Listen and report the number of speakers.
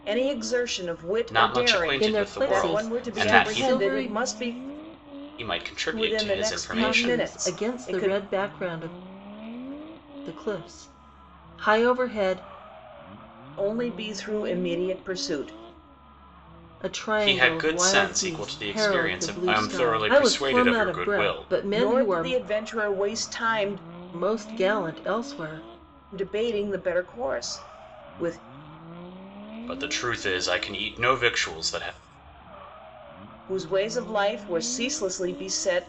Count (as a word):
three